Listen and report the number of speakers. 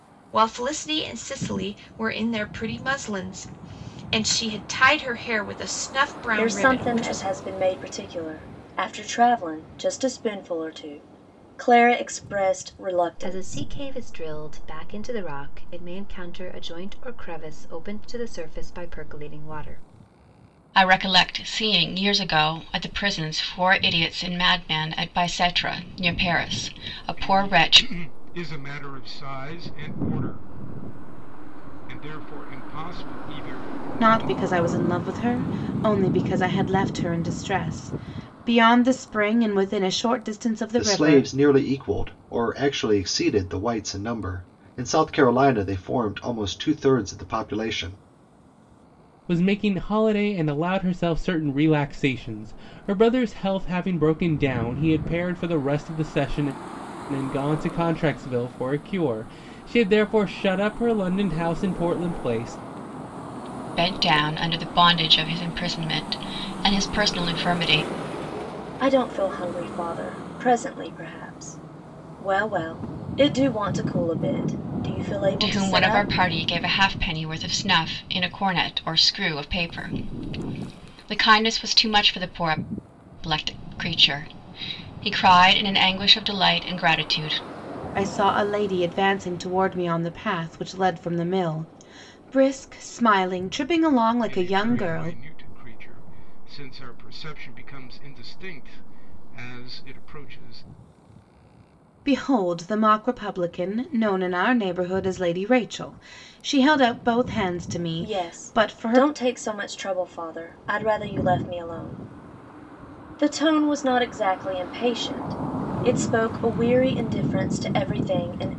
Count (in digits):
8